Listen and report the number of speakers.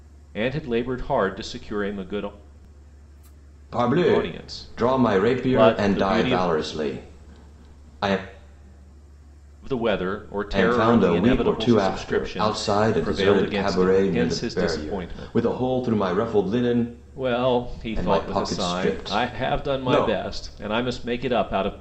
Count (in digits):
2